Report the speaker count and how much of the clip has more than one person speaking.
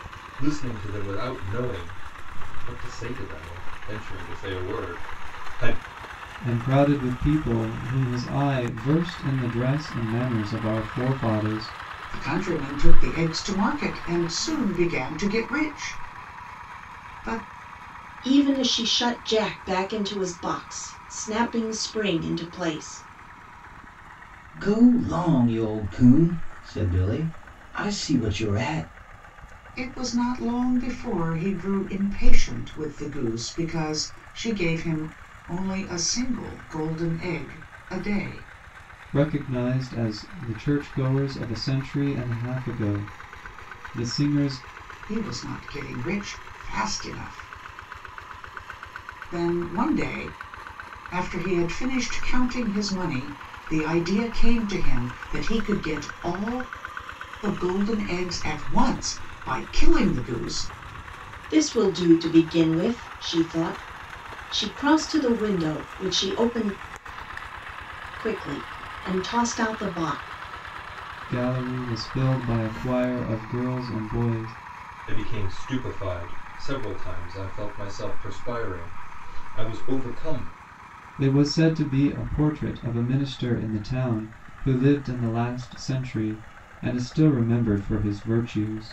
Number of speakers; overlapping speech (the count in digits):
5, no overlap